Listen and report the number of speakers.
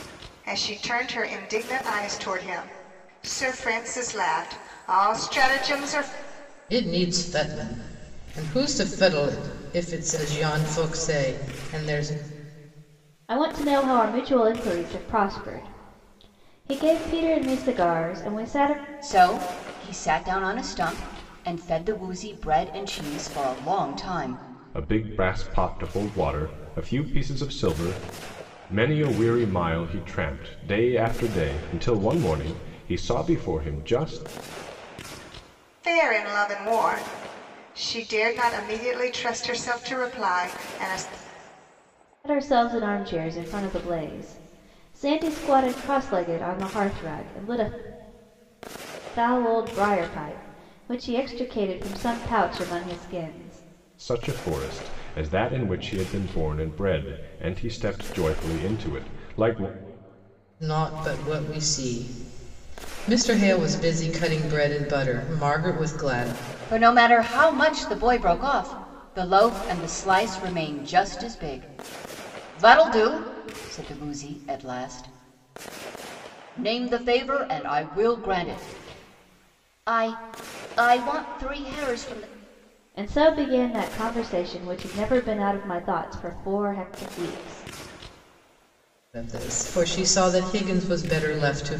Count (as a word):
five